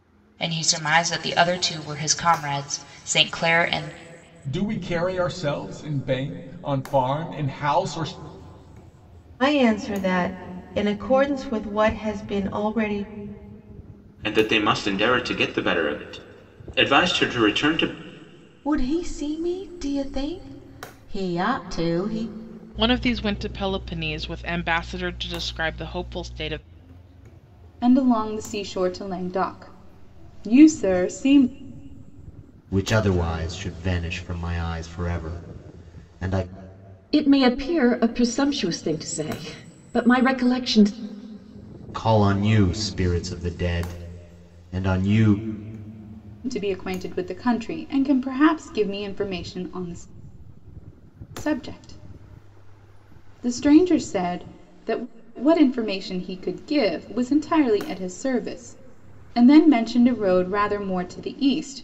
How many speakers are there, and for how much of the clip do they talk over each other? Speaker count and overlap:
9, no overlap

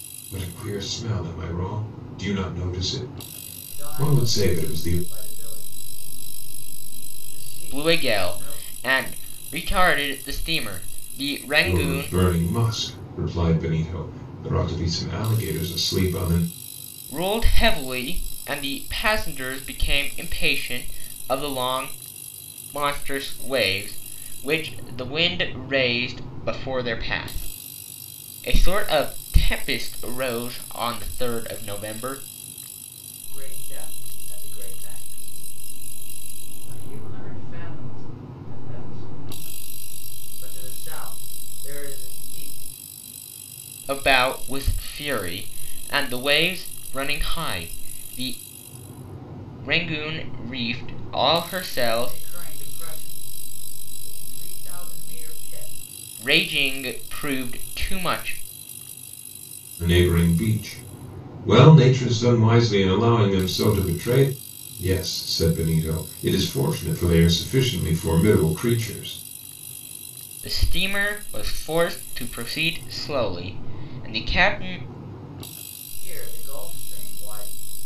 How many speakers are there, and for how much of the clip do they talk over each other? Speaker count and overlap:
3, about 4%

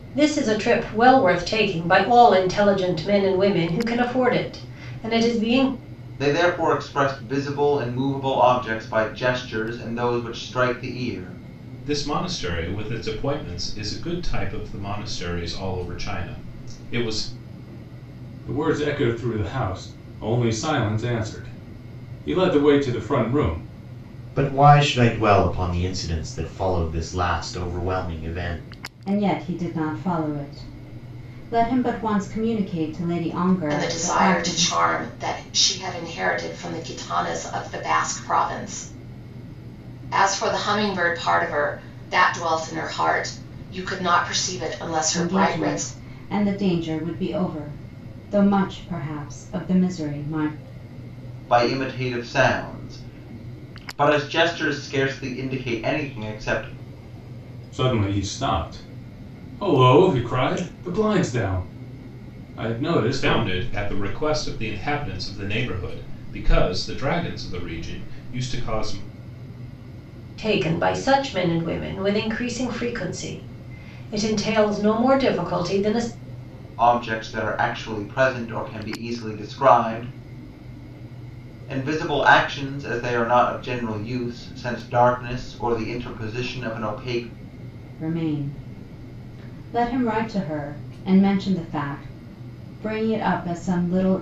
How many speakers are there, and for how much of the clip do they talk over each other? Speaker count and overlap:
7, about 2%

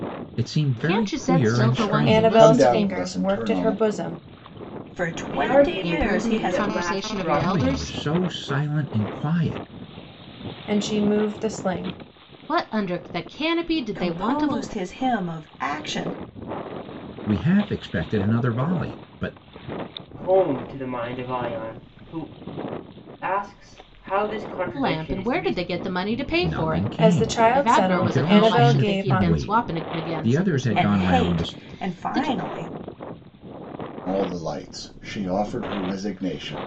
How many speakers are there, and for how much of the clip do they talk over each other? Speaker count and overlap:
6, about 36%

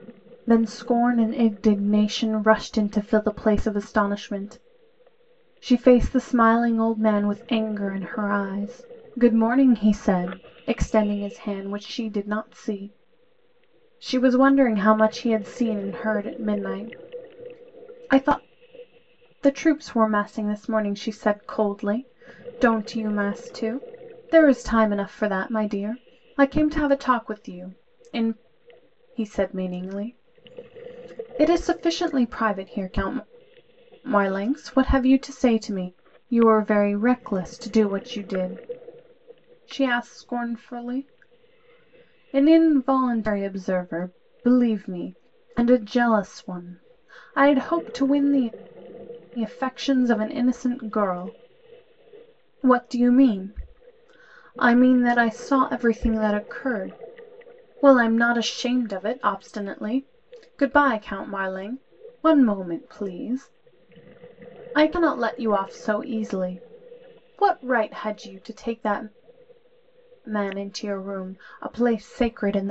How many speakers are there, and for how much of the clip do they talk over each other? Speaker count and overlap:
1, no overlap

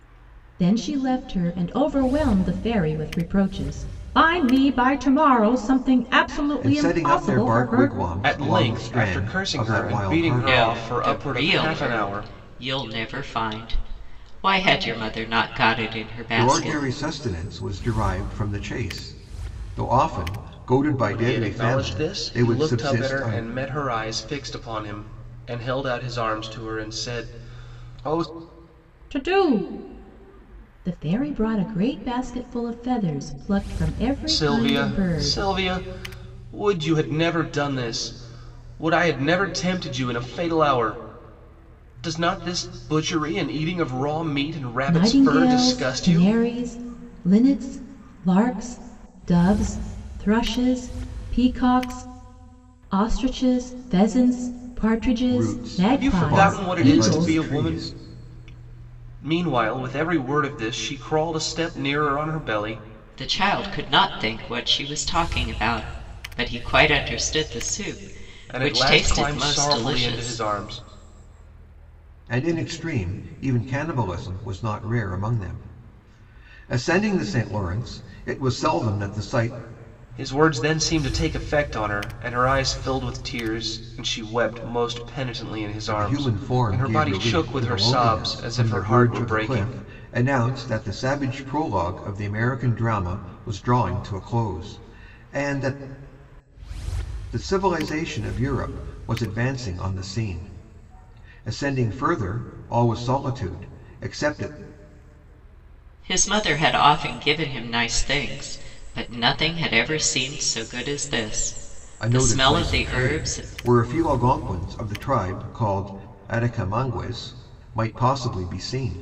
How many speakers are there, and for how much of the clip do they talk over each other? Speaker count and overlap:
4, about 18%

